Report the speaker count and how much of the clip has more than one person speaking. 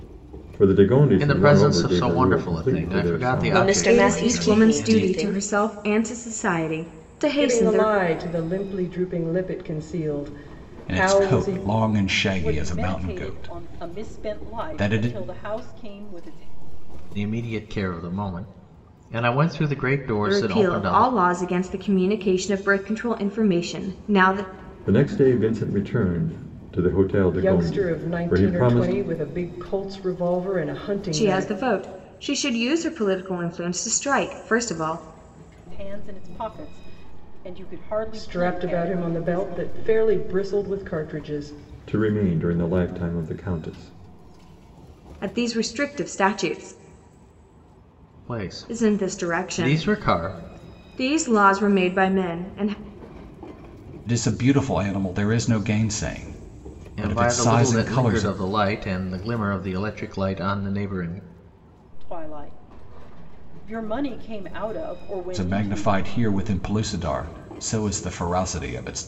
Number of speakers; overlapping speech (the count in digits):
7, about 24%